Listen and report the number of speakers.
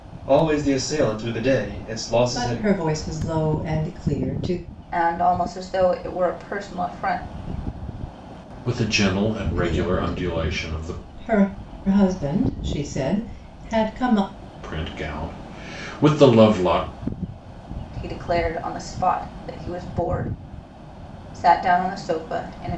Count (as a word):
four